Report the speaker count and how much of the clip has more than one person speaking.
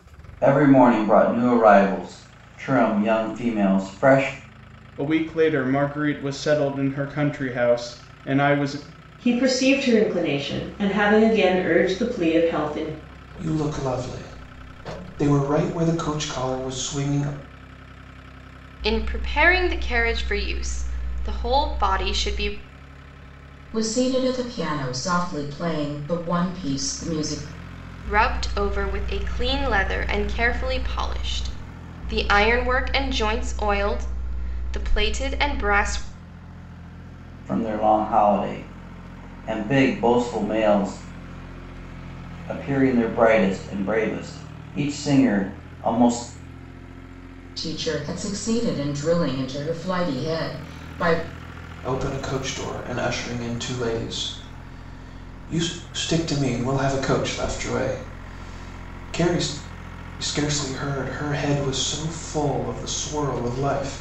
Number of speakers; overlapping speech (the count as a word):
six, no overlap